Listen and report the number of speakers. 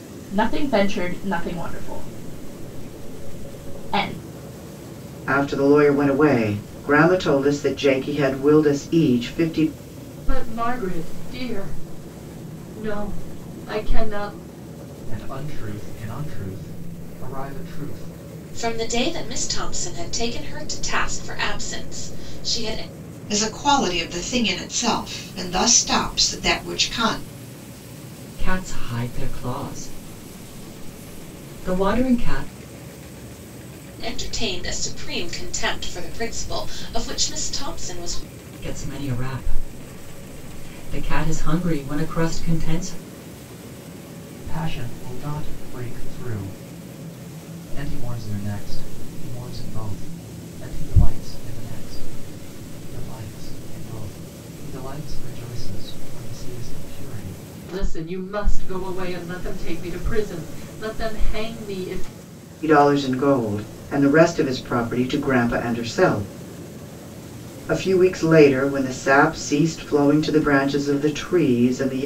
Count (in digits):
7